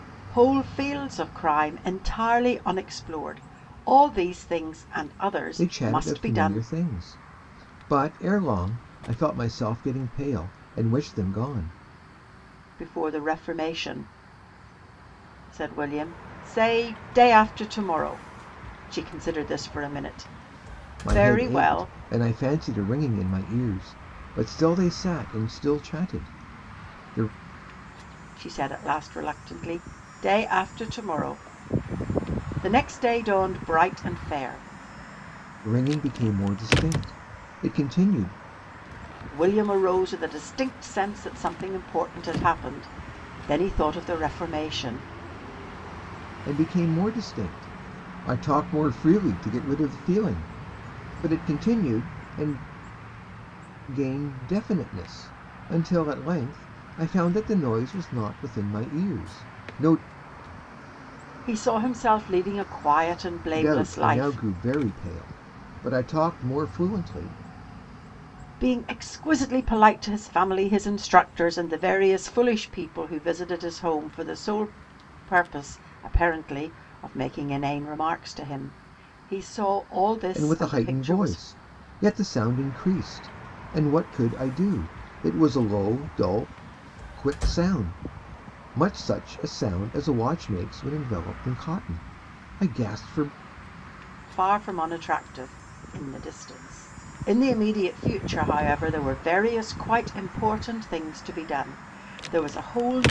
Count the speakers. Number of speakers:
2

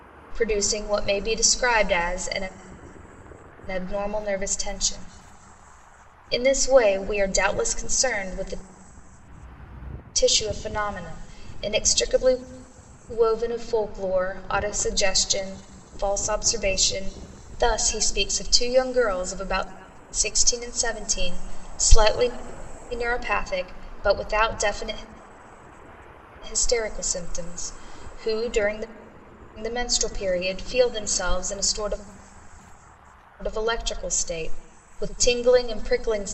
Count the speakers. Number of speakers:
1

